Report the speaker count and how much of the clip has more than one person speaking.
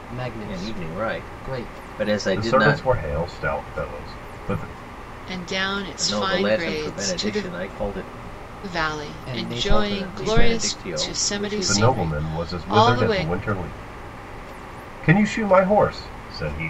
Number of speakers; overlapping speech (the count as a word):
four, about 45%